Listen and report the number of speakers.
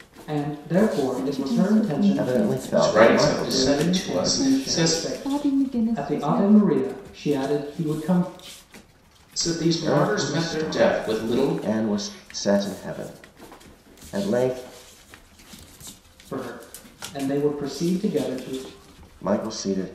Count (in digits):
4